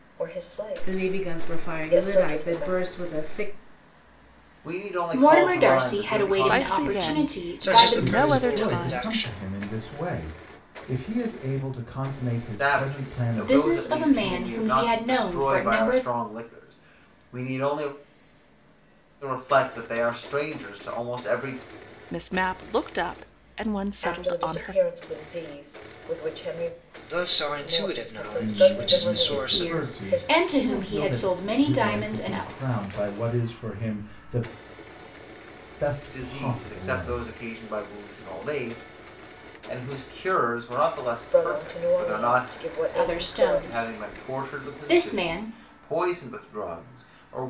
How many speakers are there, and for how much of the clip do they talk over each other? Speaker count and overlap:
7, about 44%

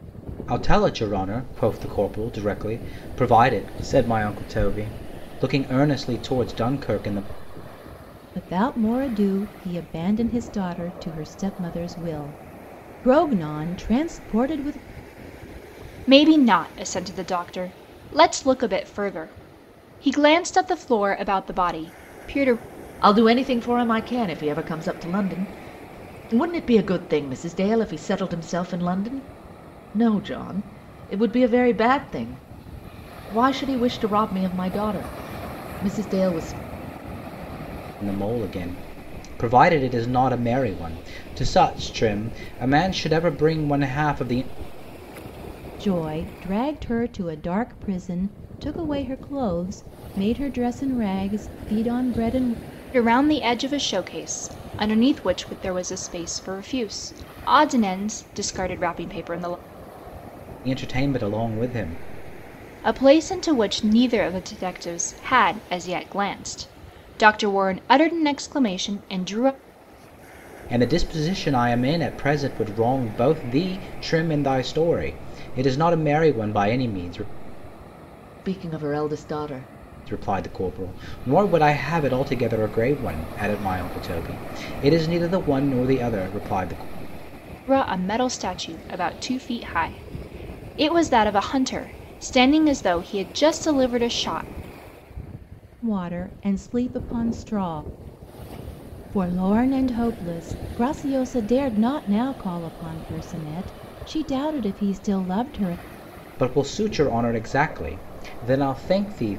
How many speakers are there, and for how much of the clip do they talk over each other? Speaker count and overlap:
4, no overlap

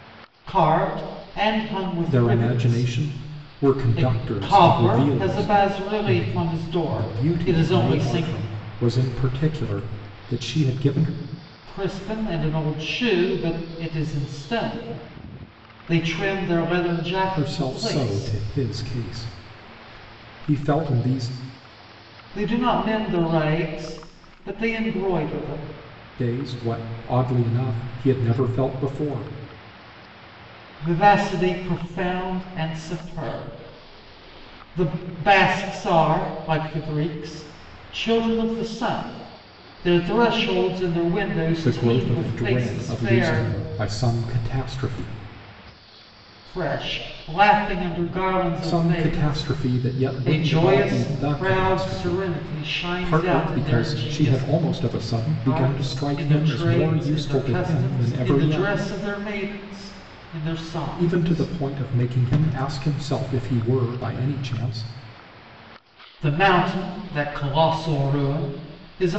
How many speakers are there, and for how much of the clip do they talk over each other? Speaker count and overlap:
2, about 25%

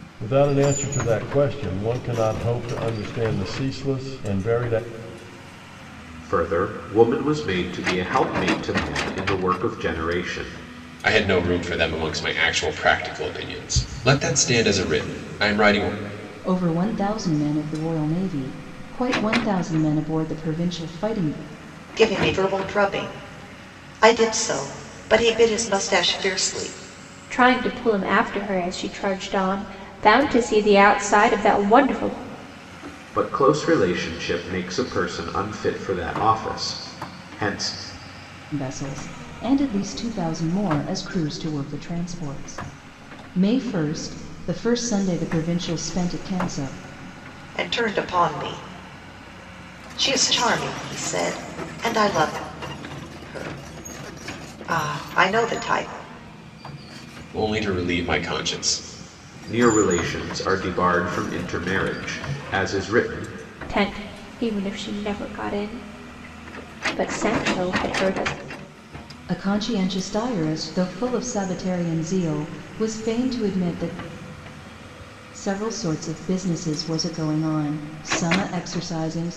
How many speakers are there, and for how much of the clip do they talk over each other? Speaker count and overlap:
6, no overlap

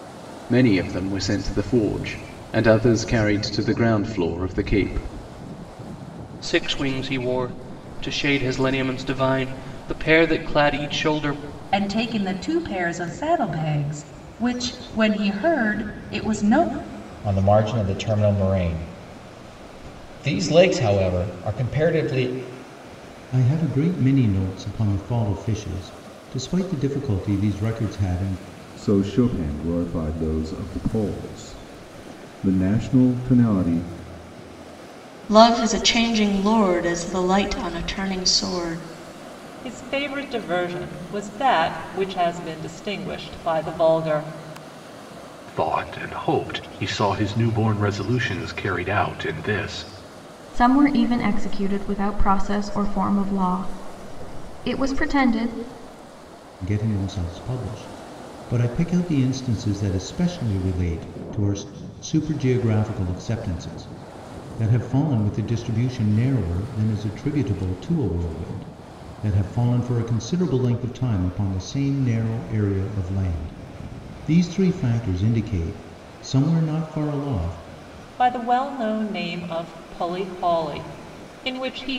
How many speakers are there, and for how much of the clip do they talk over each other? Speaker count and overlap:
10, no overlap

